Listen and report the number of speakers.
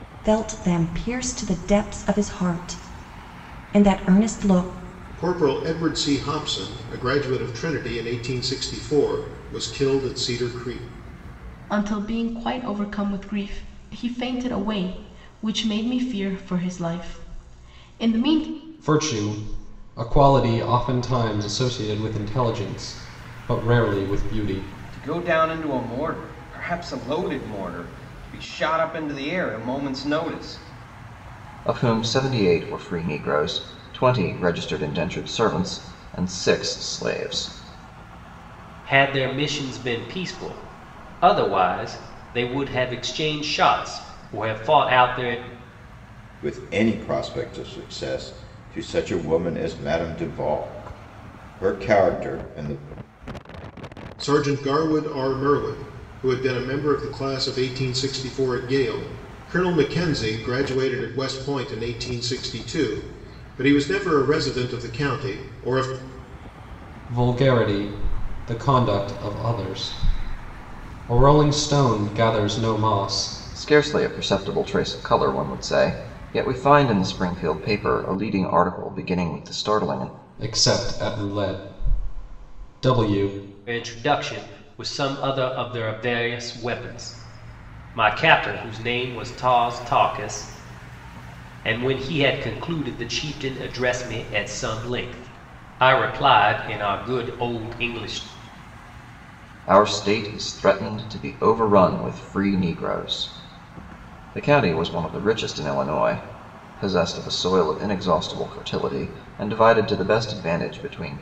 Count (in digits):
8